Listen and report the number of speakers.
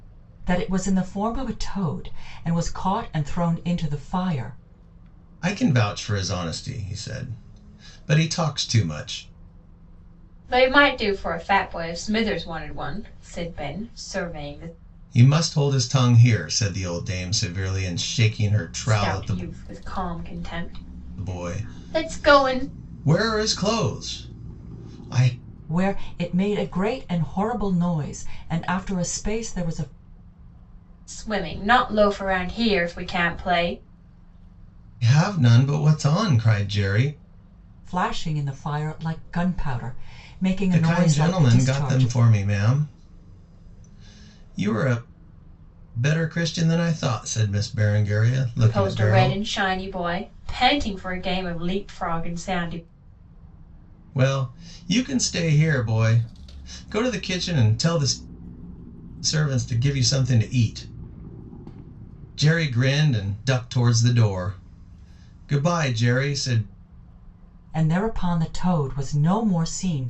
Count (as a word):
three